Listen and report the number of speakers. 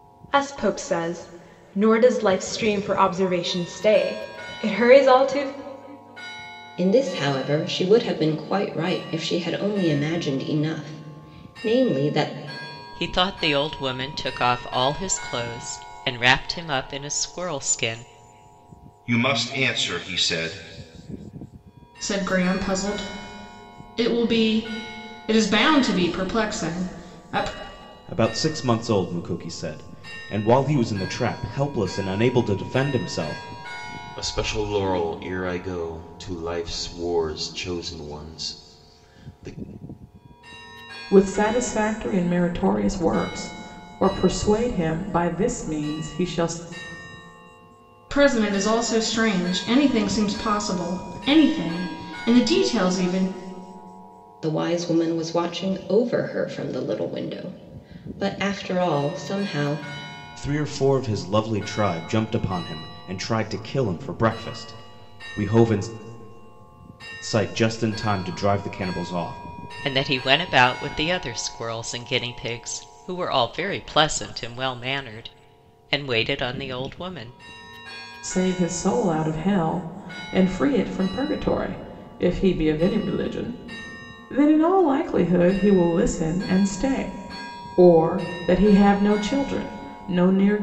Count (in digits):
8